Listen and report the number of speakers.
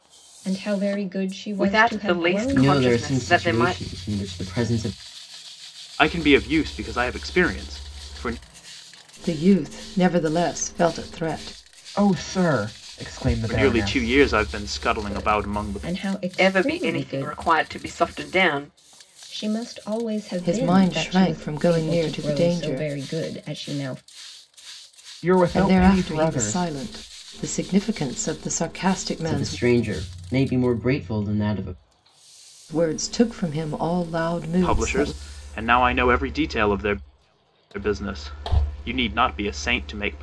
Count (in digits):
6